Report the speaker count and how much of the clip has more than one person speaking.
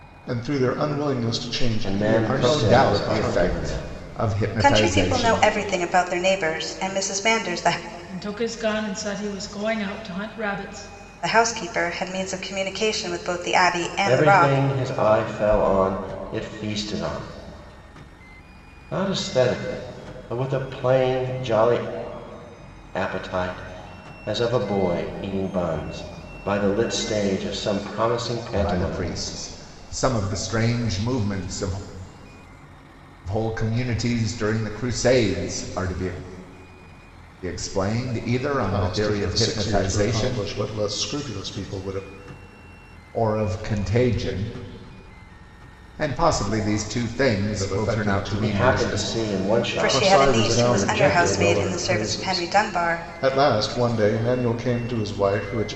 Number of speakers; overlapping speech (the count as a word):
five, about 21%